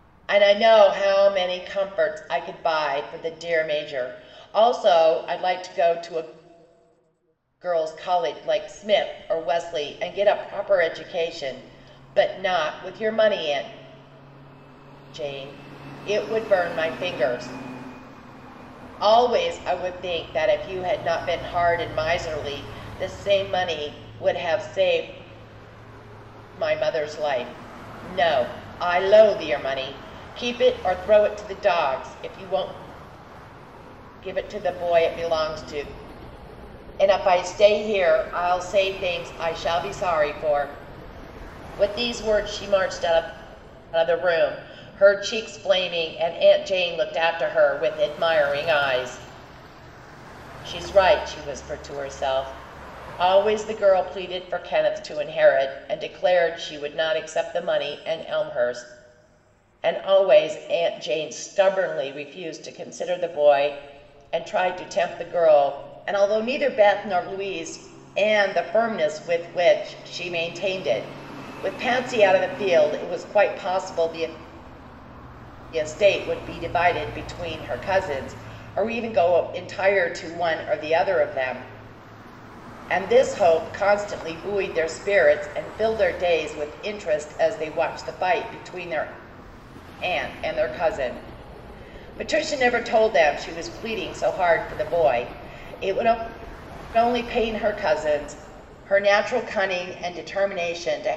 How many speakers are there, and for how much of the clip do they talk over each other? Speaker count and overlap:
1, no overlap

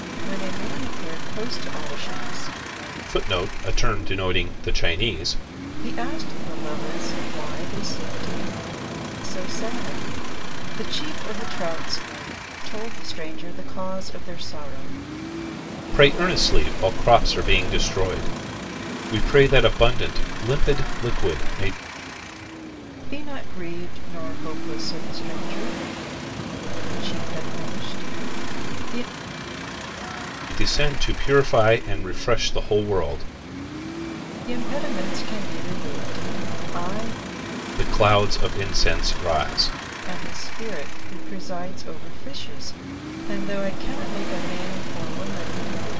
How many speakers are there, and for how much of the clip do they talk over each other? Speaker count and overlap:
2, no overlap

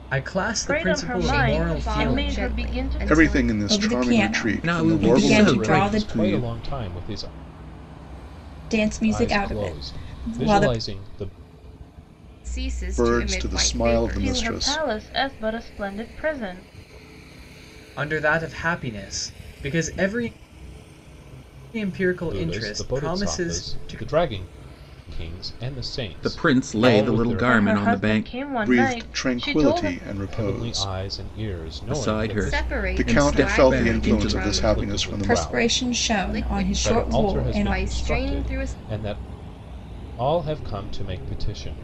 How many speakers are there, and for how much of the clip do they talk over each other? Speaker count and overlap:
7, about 52%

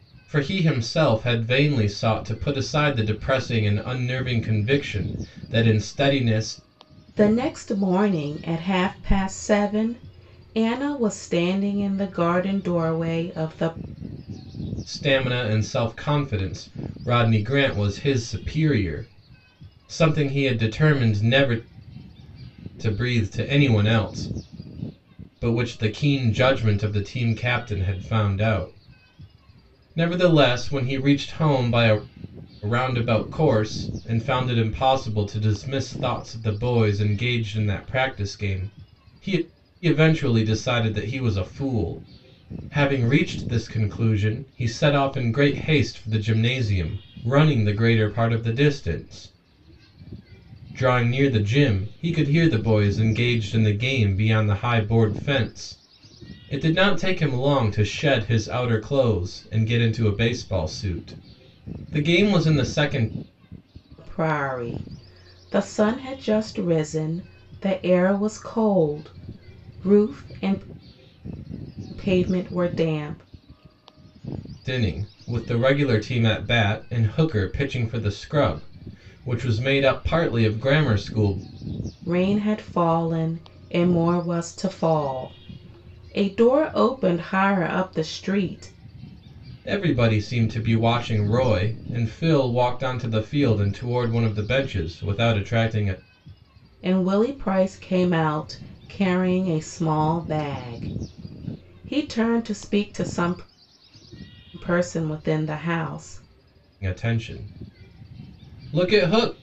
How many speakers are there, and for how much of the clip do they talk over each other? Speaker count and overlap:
2, no overlap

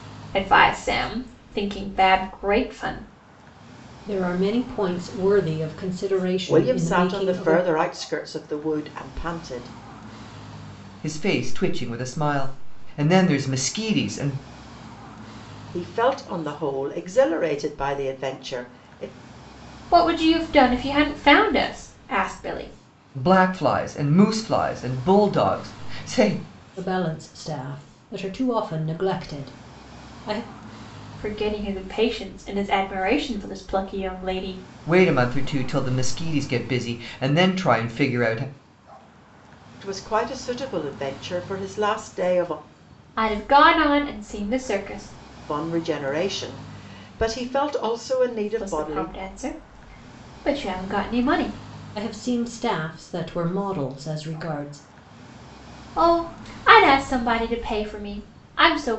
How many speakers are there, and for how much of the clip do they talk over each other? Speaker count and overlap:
4, about 3%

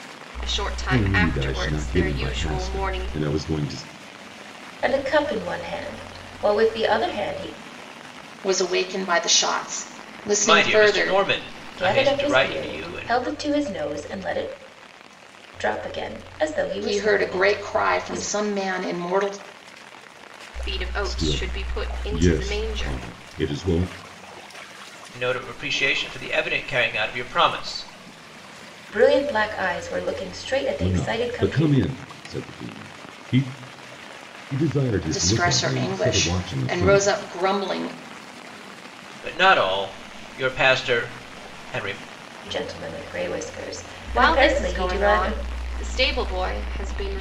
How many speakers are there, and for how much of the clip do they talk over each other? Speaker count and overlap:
5, about 26%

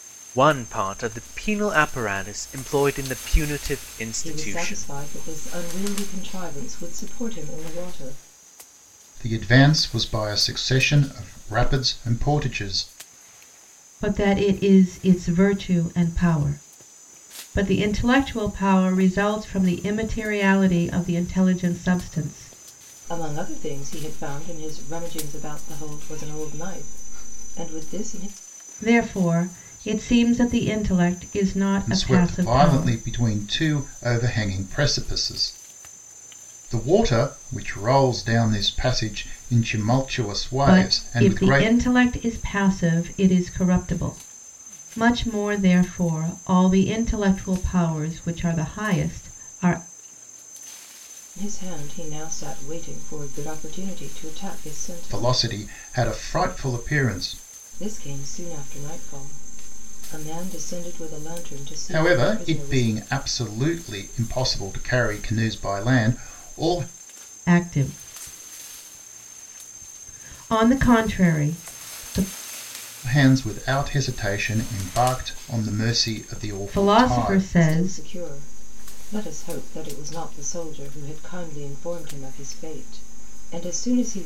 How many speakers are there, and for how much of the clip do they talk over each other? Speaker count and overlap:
4, about 7%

